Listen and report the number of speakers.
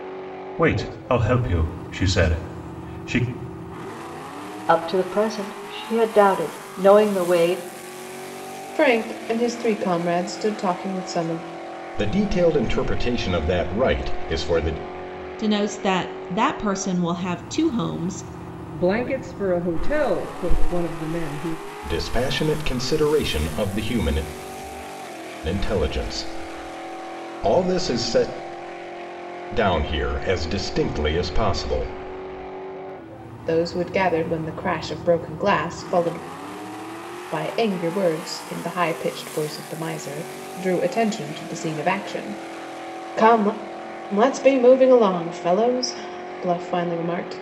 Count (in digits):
6